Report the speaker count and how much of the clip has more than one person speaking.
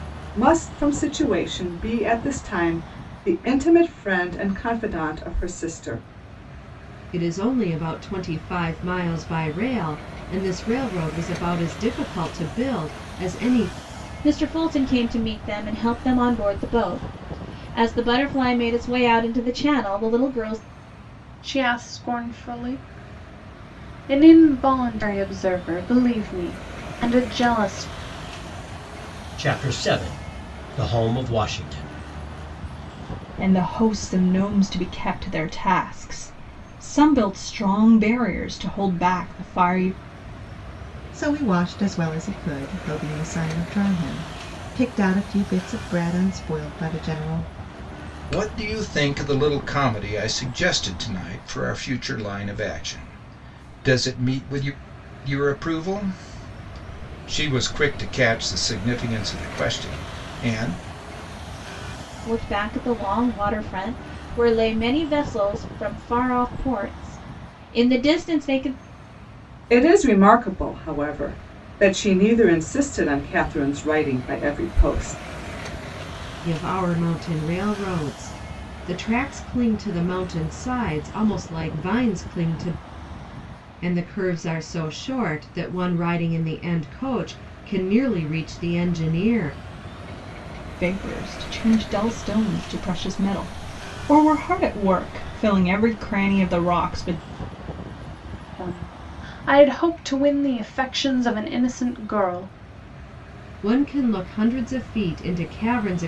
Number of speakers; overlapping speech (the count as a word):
eight, no overlap